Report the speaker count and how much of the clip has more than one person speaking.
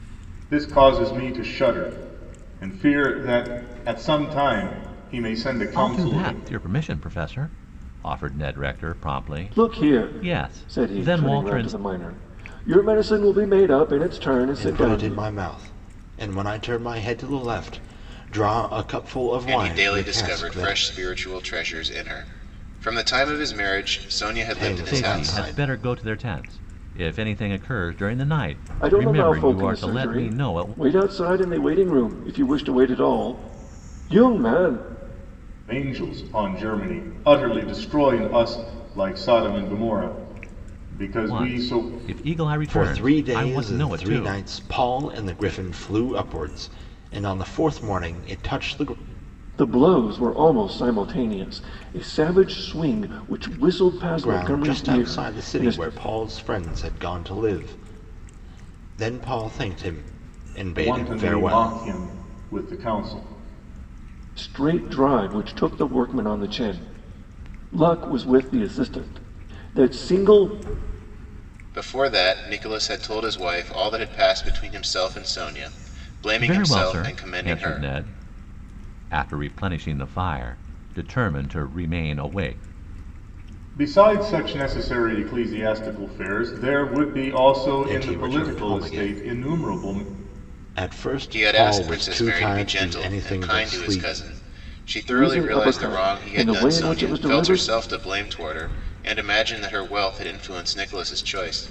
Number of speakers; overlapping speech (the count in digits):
5, about 22%